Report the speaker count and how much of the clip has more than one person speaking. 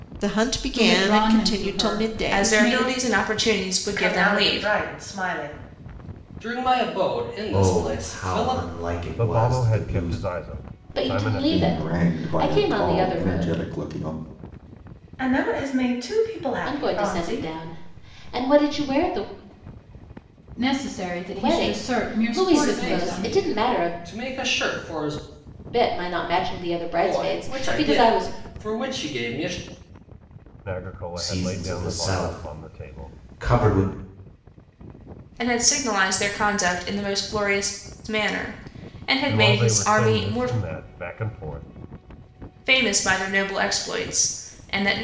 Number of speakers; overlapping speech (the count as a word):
nine, about 37%